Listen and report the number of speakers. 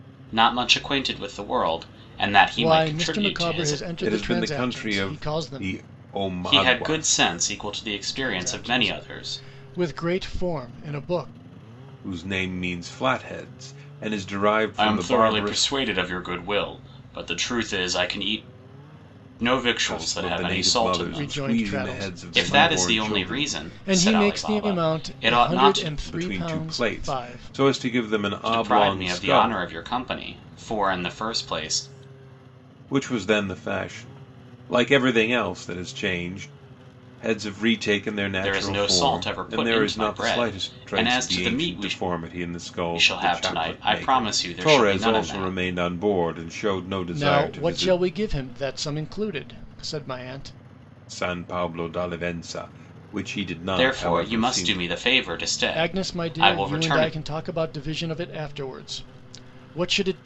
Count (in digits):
3